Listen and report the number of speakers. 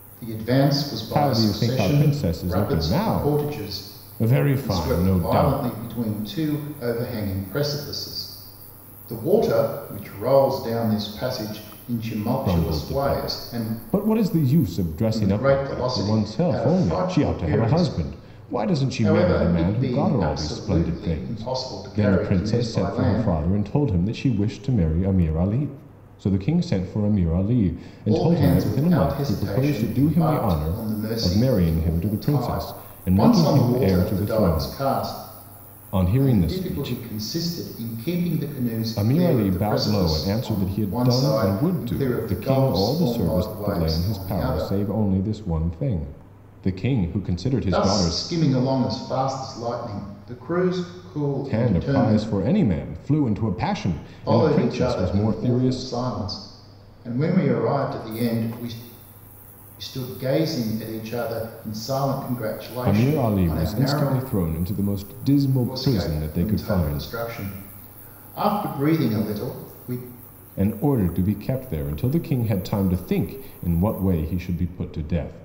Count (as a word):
two